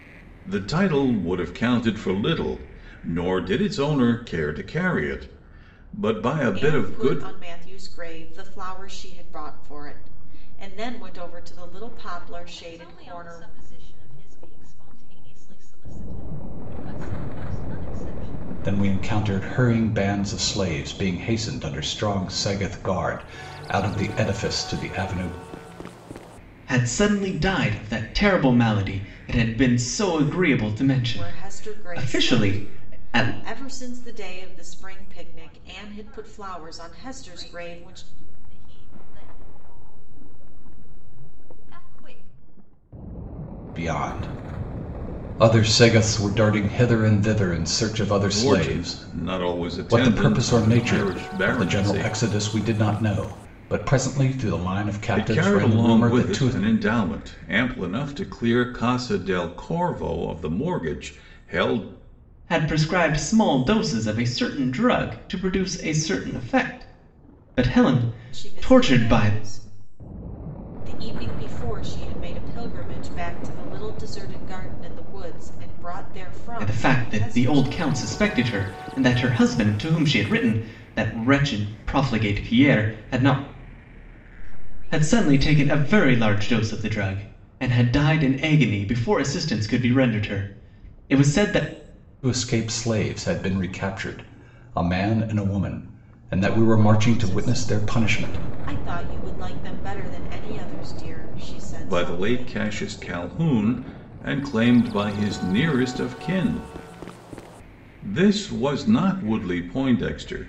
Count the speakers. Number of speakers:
5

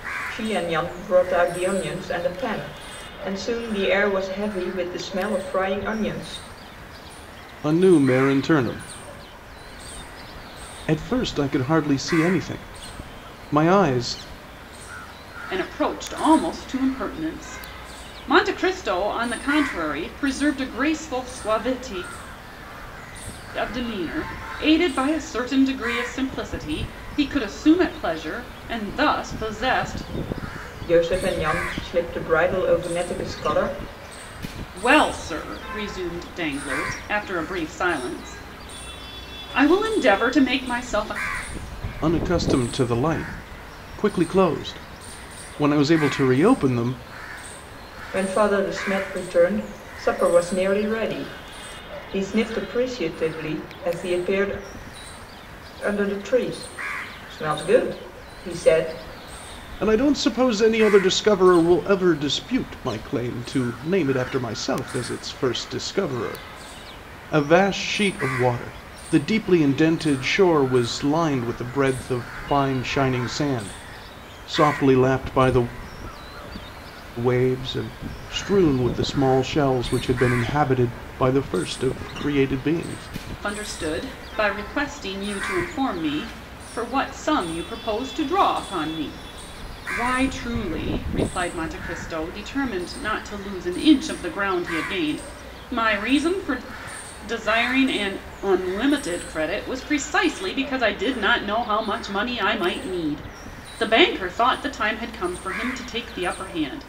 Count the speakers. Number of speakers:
3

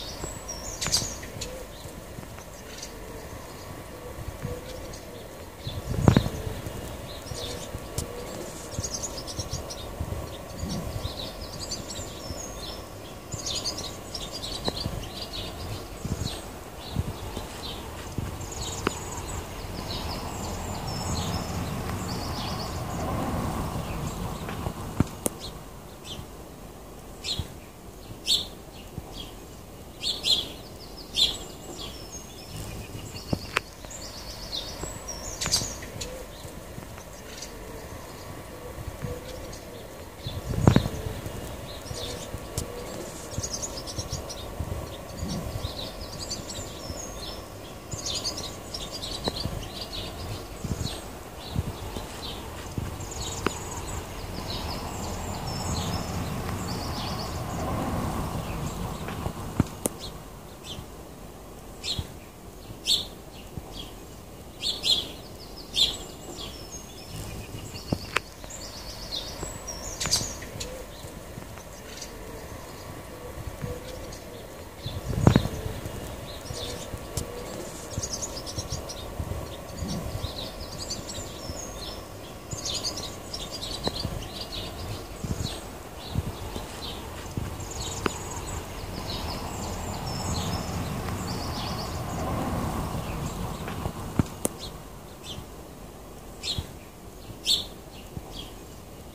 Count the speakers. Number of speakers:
0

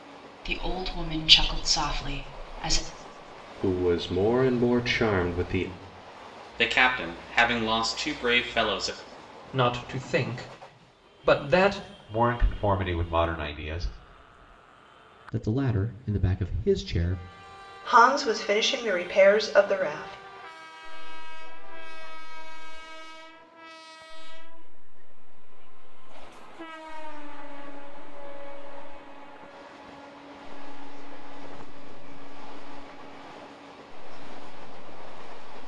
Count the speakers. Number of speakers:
8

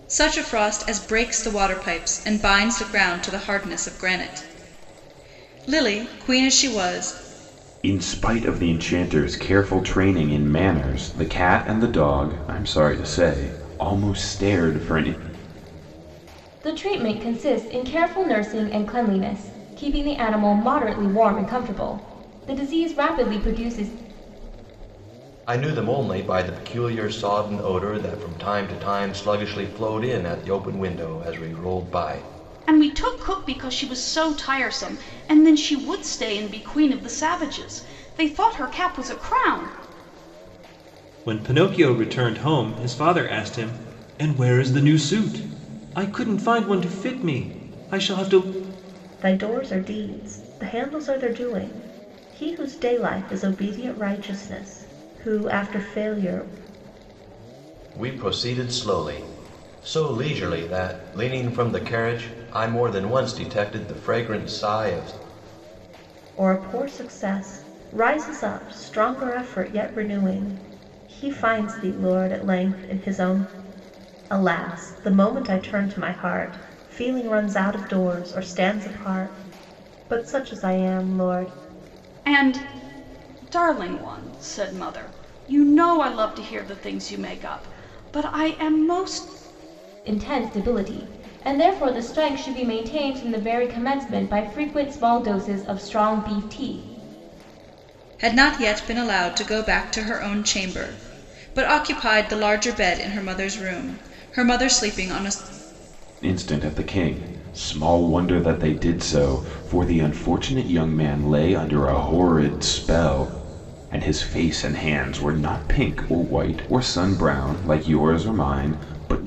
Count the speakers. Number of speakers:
7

